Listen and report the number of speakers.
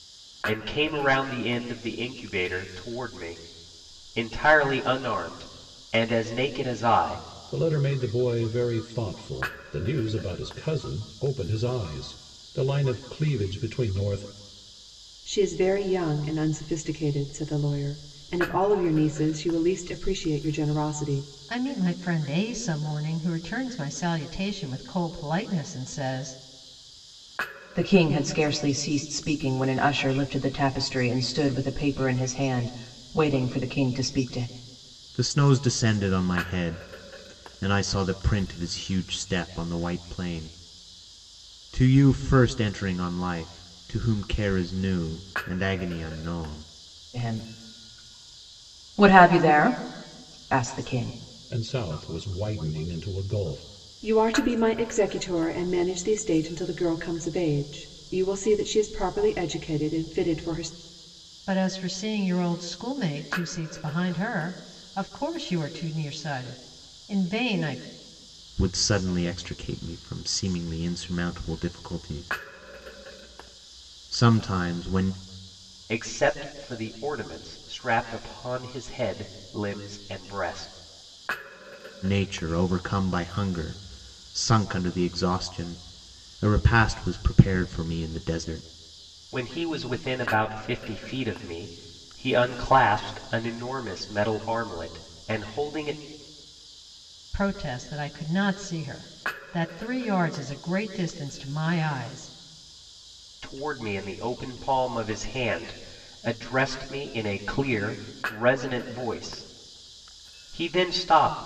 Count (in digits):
6